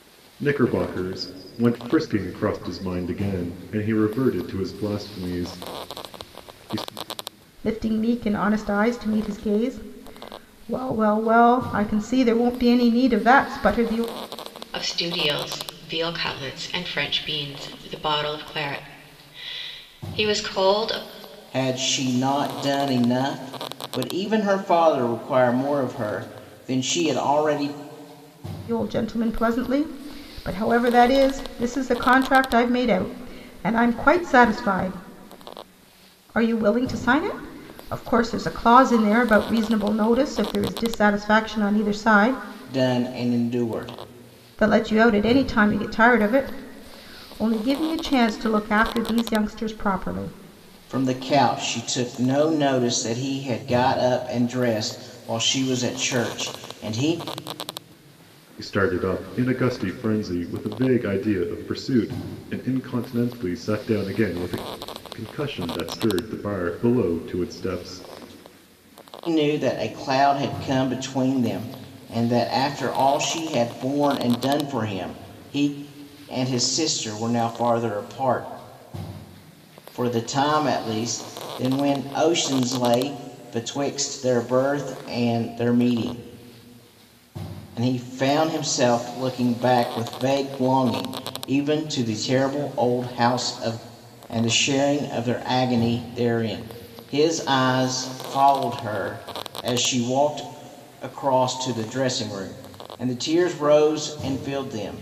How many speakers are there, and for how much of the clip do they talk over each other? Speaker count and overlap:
4, no overlap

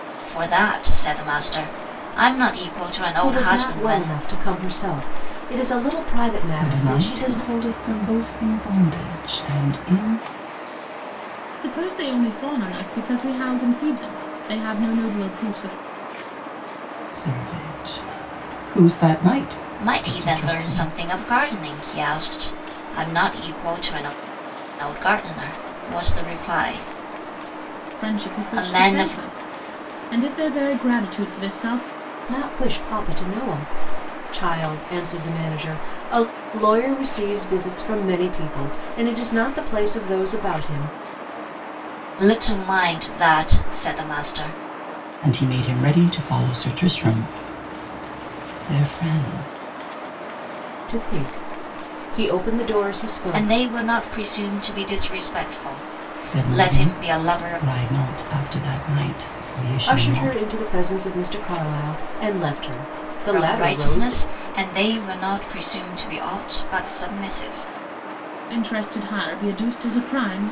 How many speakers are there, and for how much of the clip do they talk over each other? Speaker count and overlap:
4, about 11%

